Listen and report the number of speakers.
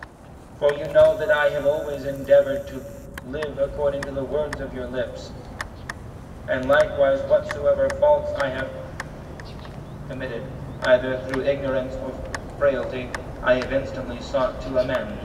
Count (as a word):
one